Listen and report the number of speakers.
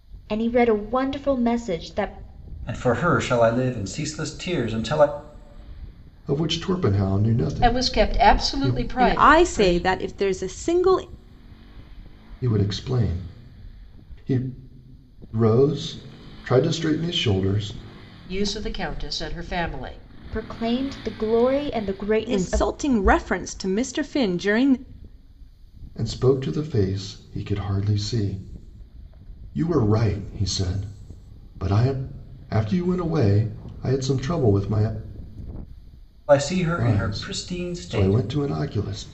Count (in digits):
5